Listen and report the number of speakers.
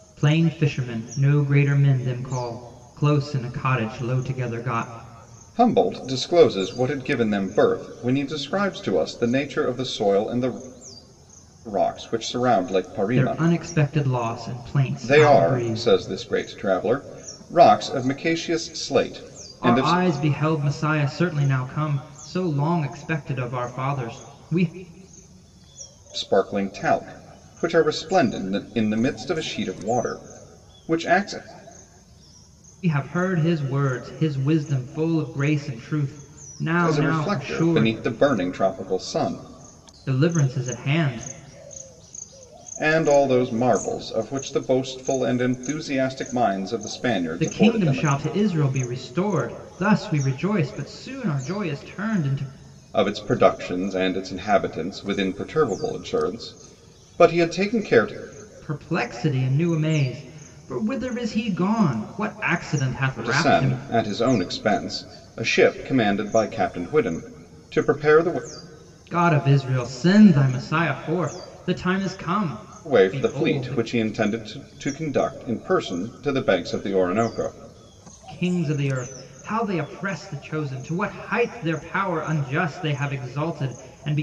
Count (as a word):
two